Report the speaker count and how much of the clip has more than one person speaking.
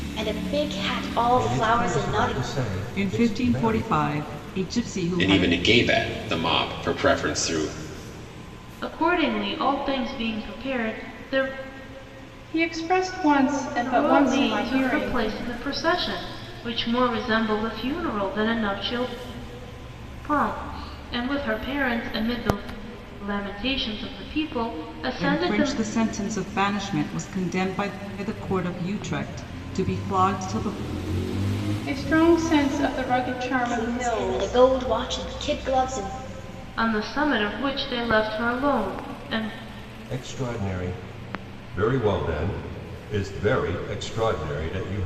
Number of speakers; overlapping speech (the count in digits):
6, about 12%